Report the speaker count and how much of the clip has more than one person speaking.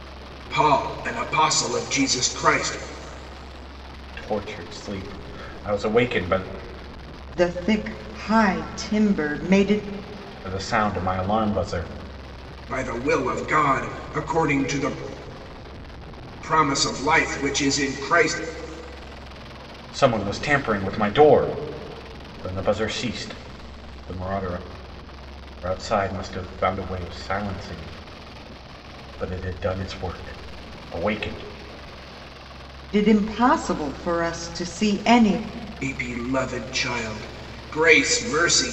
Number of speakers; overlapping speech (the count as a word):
three, no overlap